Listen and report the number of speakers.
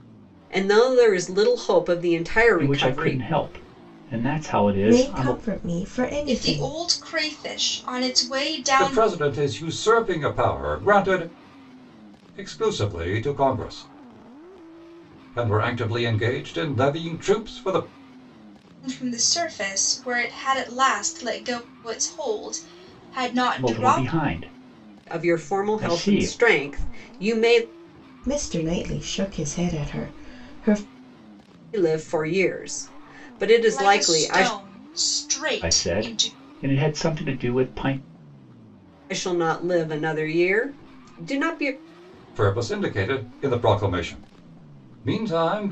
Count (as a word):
five